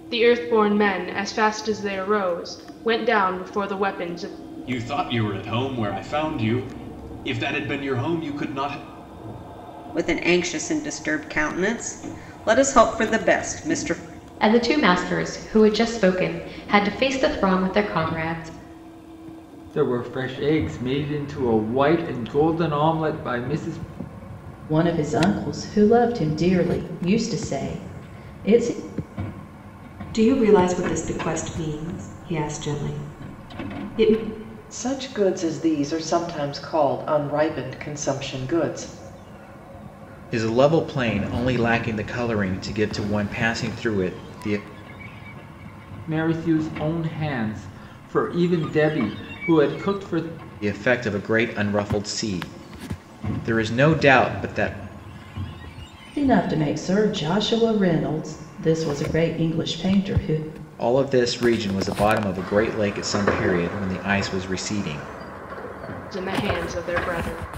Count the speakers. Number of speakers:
9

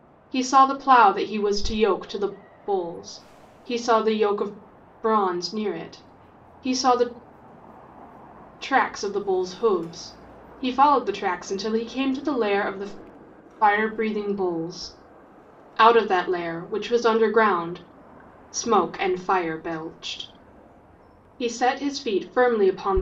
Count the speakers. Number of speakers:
1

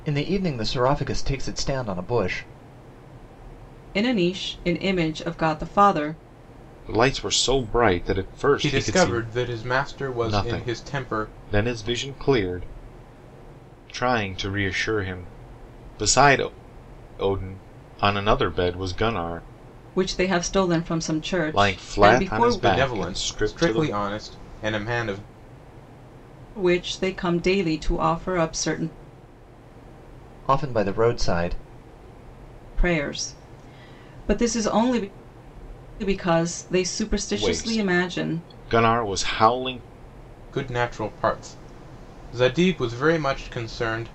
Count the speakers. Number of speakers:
4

